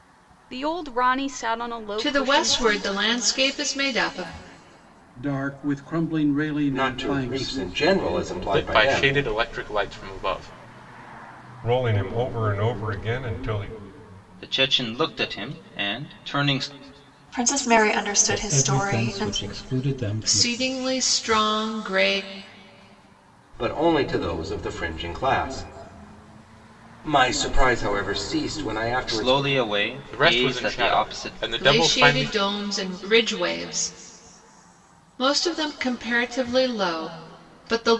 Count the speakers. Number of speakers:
9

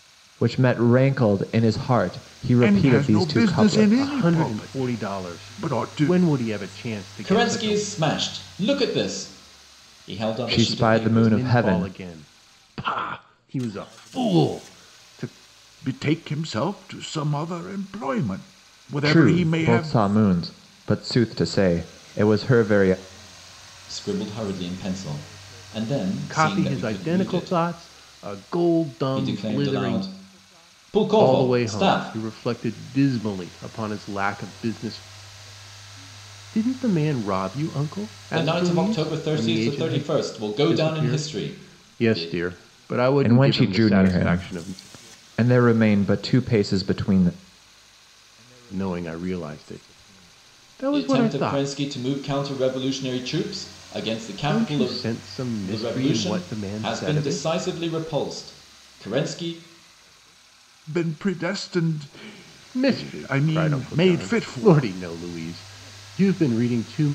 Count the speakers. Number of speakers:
4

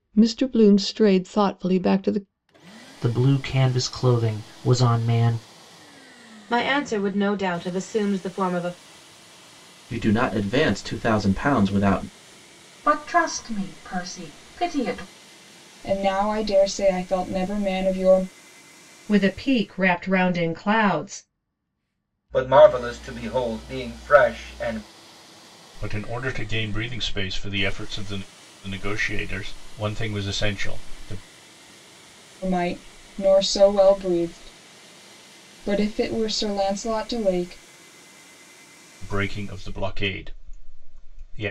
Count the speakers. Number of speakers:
9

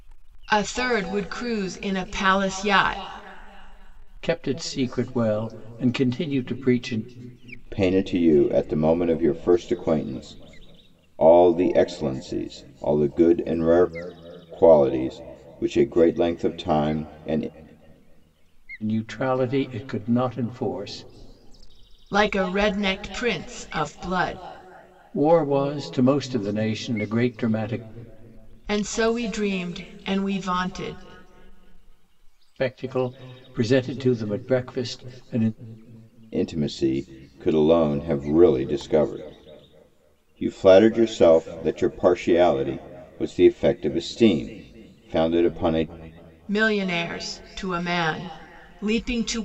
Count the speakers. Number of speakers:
3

